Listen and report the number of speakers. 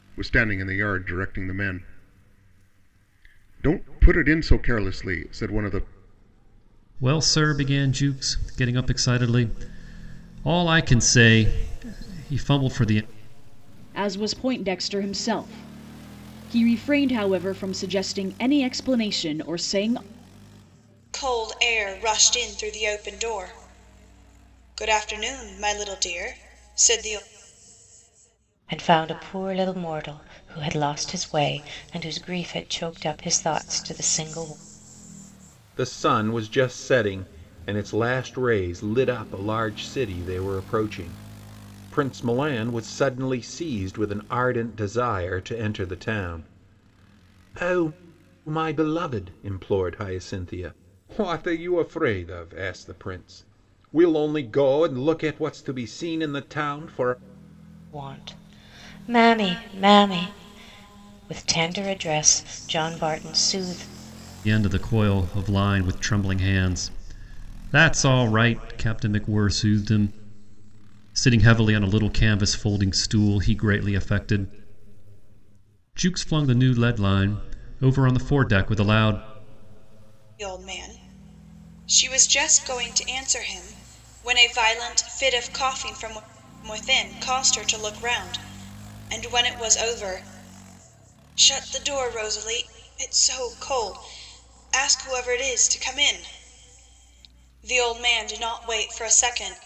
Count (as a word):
six